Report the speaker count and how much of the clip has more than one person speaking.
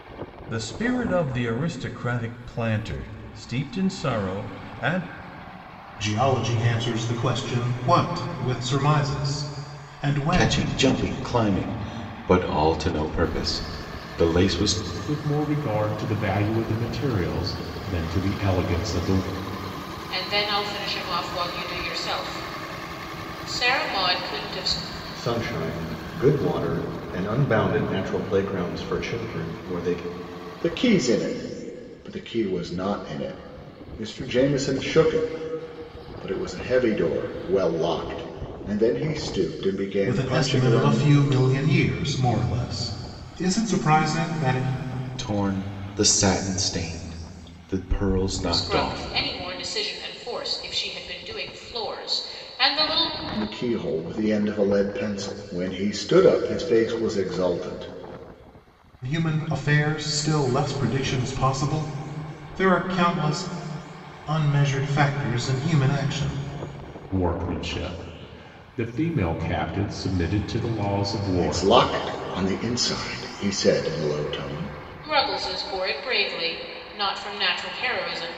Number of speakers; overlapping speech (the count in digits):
7, about 3%